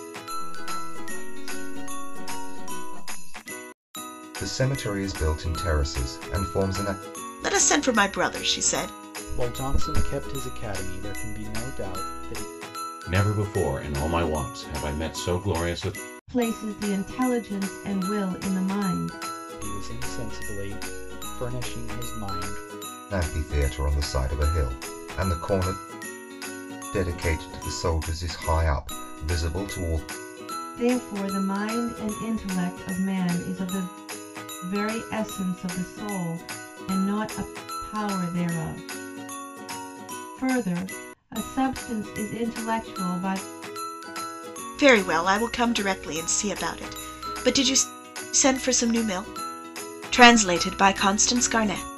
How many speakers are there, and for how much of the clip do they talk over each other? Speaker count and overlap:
6, no overlap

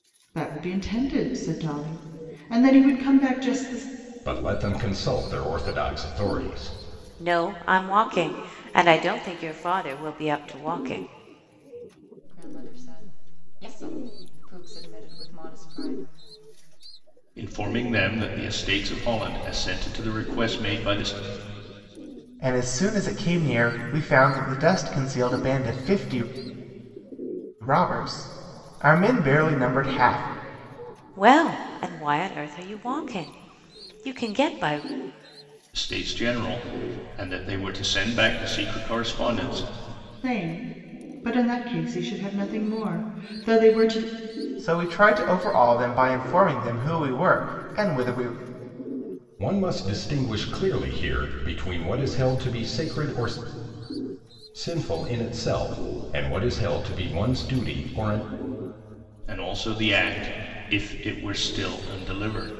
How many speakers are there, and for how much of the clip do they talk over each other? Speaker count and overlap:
6, no overlap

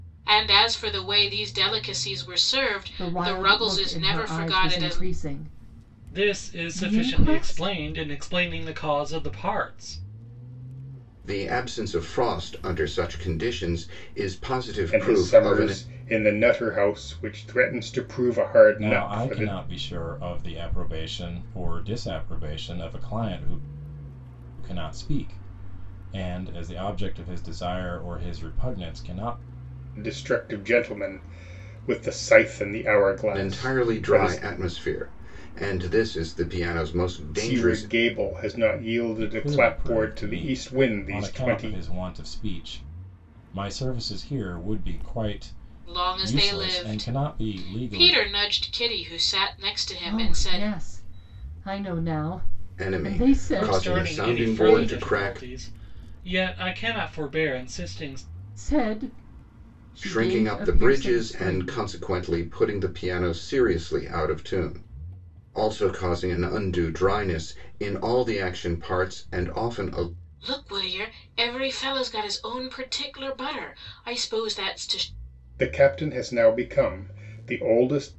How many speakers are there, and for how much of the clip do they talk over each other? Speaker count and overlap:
6, about 22%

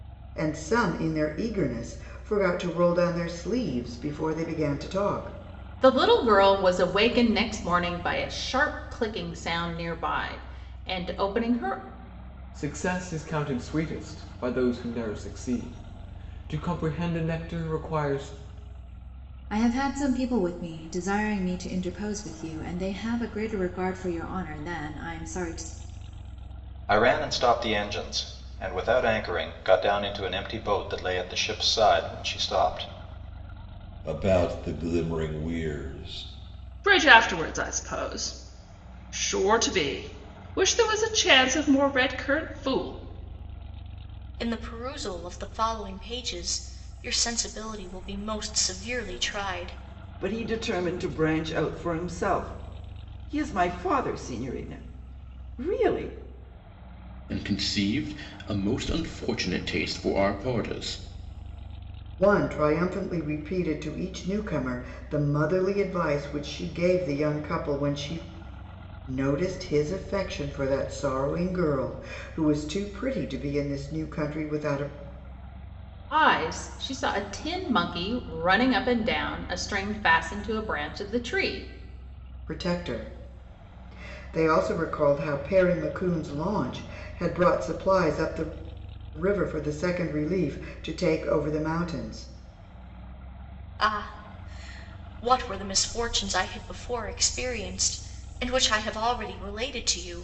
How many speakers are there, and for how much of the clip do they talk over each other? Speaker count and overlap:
10, no overlap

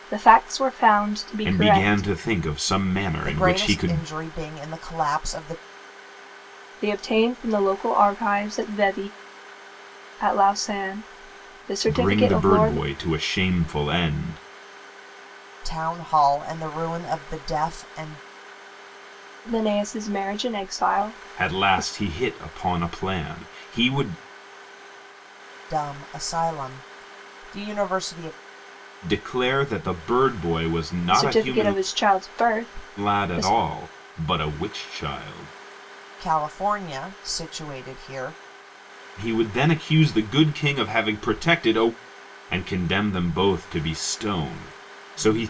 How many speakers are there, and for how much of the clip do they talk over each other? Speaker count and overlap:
3, about 9%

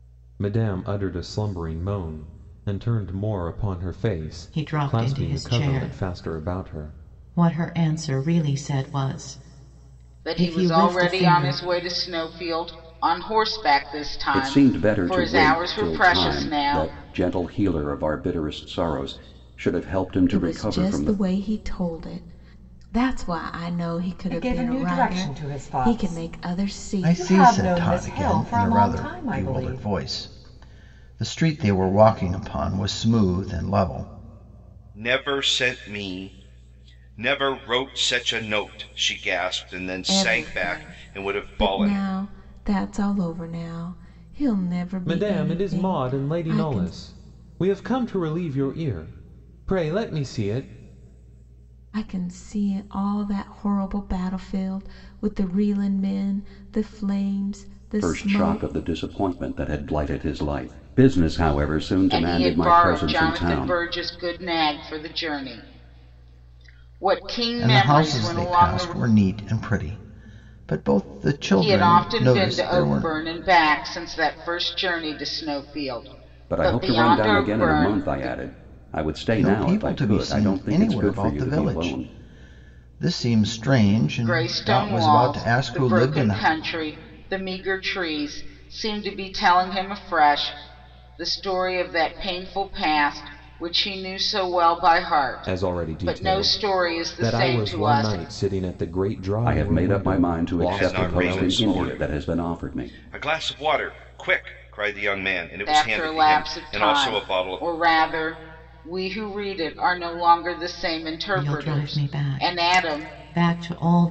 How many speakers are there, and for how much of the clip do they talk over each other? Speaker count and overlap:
8, about 35%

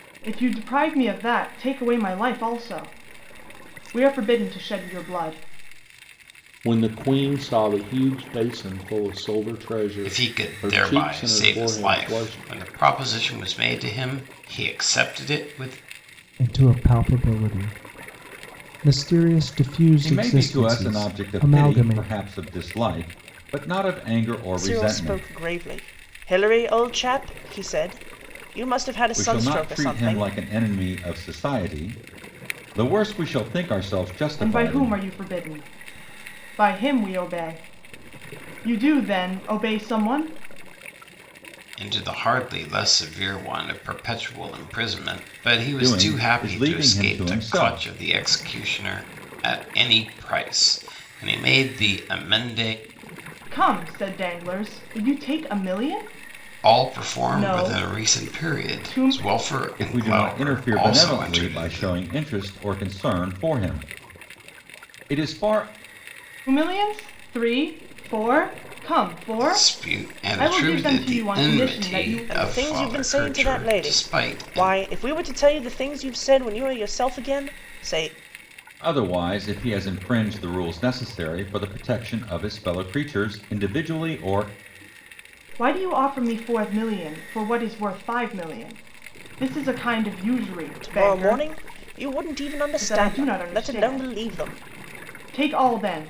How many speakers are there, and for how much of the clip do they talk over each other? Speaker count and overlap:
6, about 23%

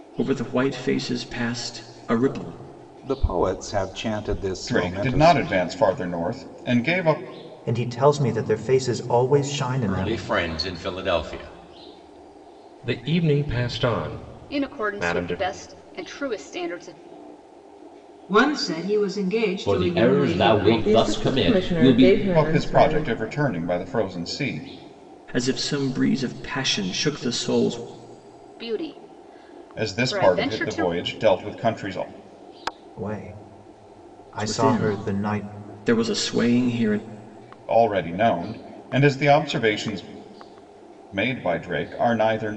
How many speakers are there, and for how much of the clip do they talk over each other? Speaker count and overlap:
10, about 18%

